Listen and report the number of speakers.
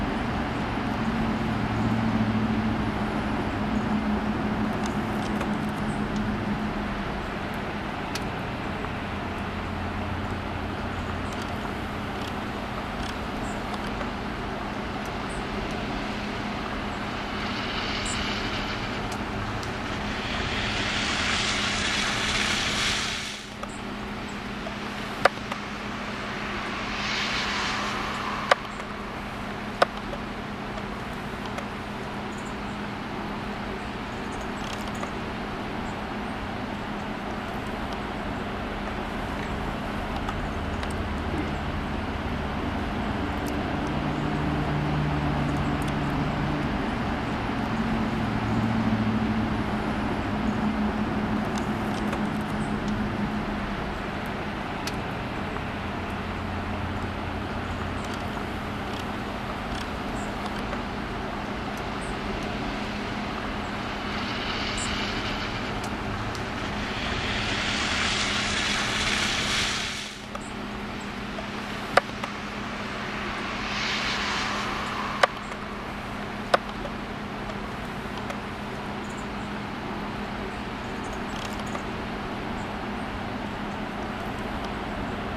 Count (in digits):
0